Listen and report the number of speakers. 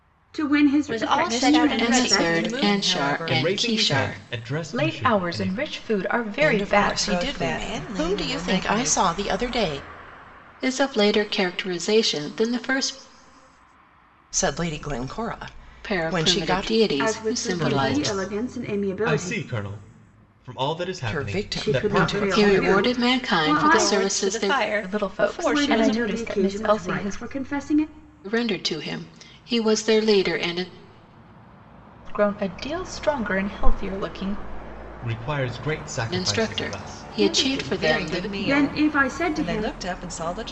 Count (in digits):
7